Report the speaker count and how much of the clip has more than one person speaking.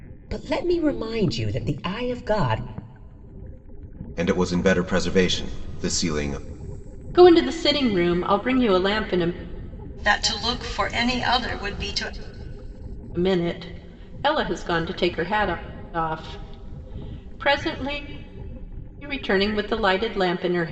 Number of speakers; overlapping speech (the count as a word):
four, no overlap